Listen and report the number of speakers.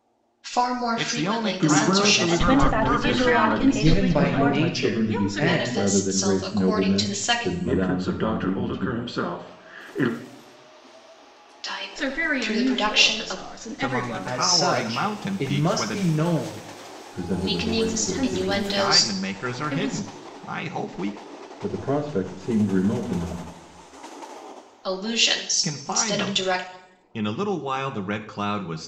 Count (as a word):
seven